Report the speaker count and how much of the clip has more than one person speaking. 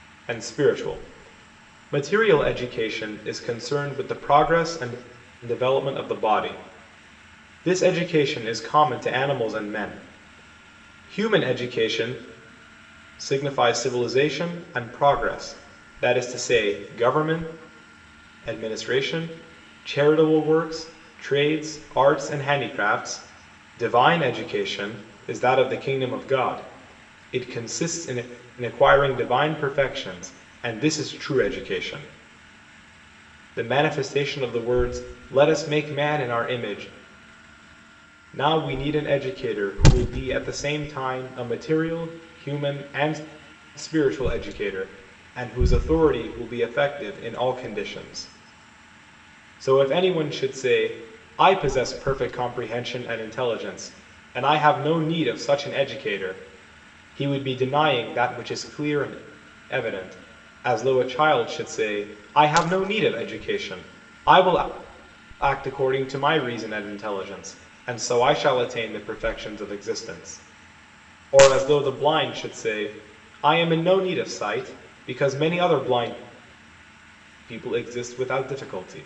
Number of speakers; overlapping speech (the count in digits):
1, no overlap